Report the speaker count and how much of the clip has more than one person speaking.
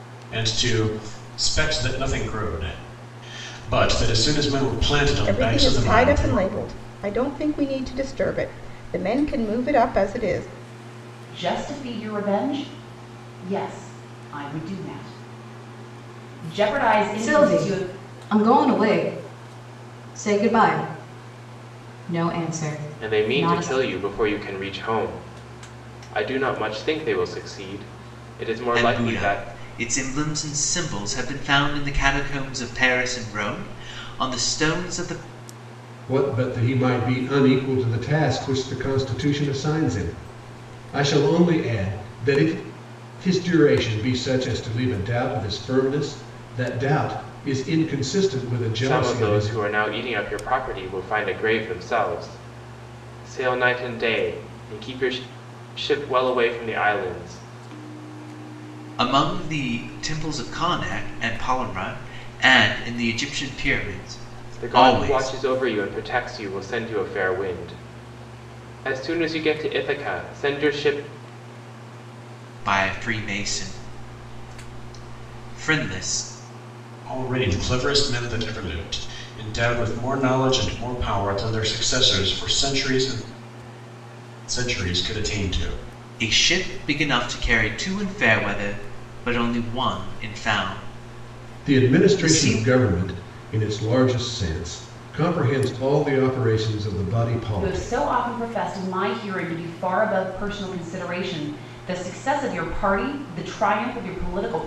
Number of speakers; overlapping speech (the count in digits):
7, about 6%